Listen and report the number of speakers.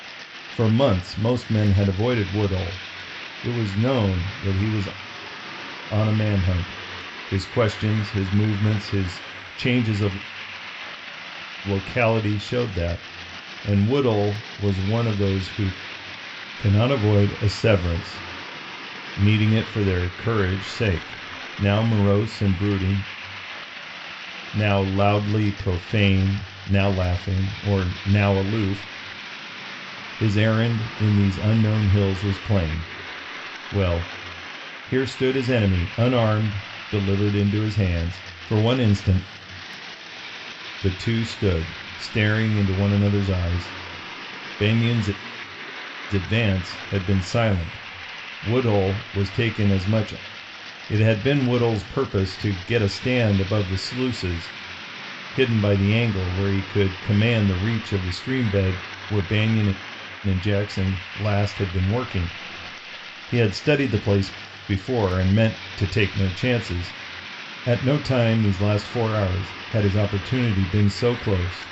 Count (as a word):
one